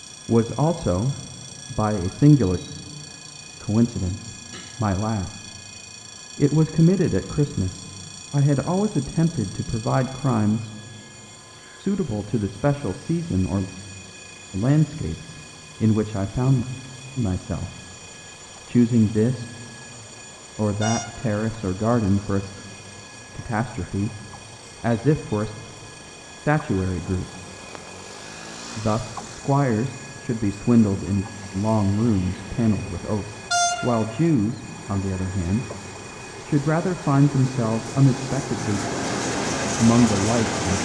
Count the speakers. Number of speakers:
1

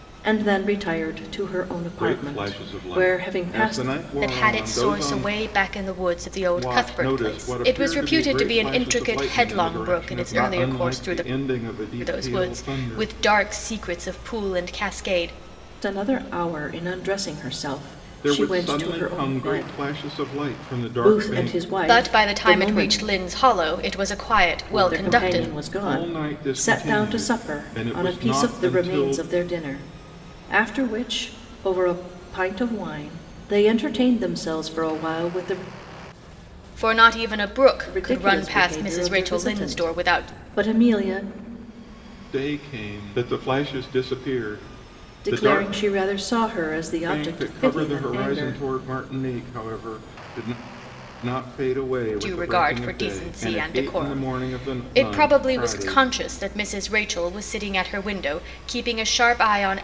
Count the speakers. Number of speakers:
3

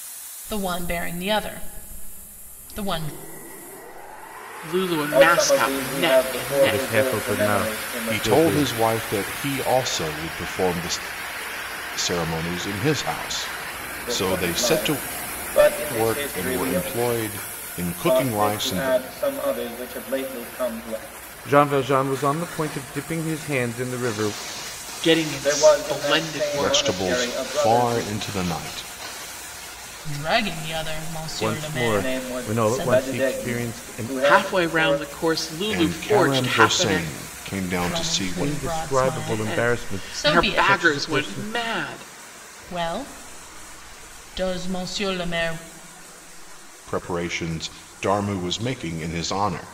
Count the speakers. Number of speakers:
5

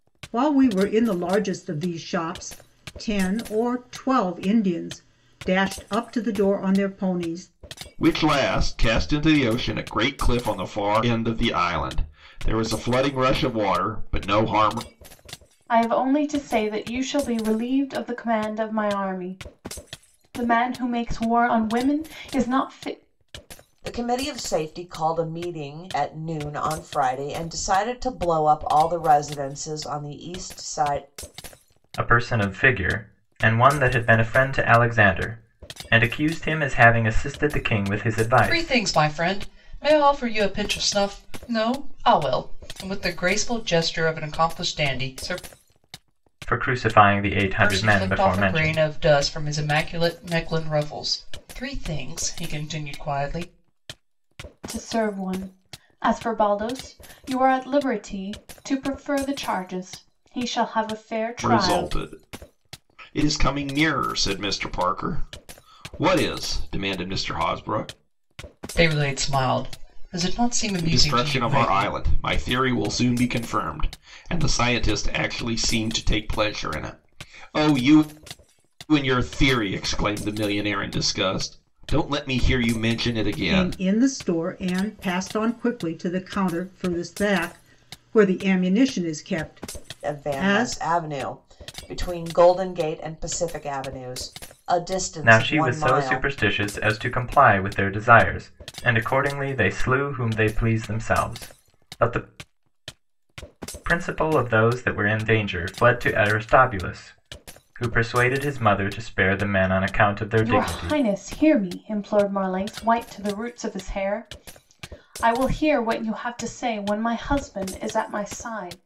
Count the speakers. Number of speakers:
6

